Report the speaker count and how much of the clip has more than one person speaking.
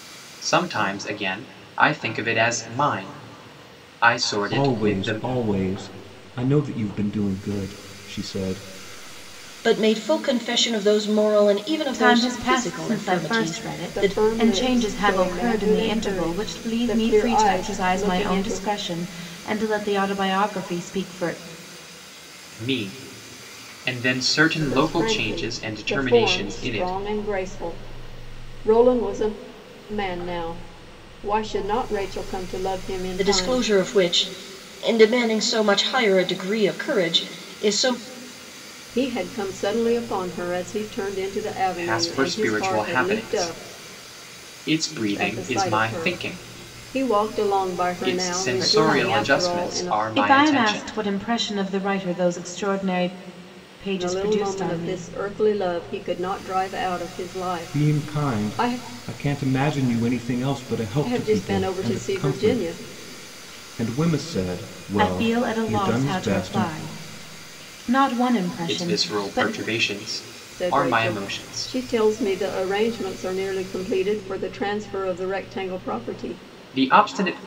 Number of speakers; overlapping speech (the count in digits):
5, about 31%